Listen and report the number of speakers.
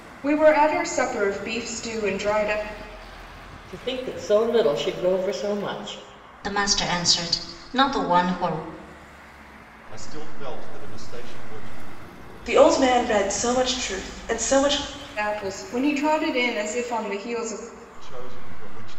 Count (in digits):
5